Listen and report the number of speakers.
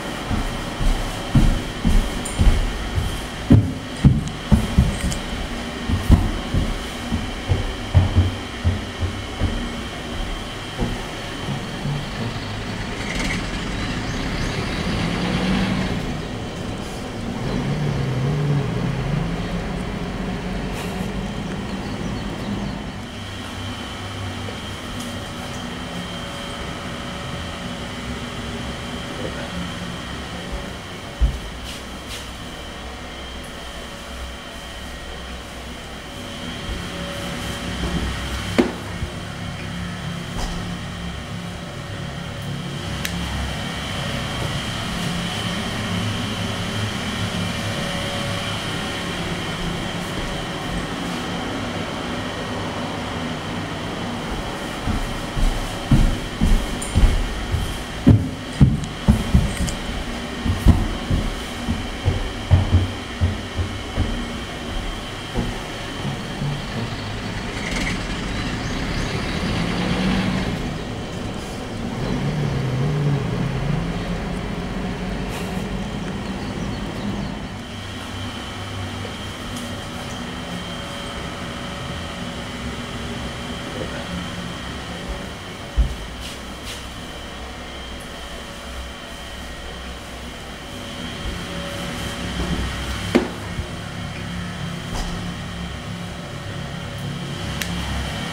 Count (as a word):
zero